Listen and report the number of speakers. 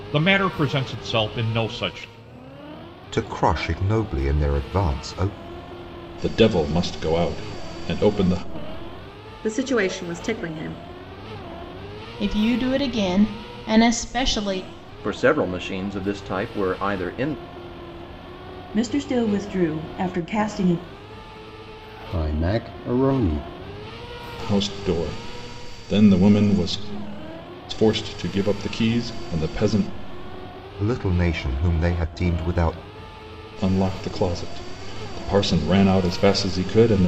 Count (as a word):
eight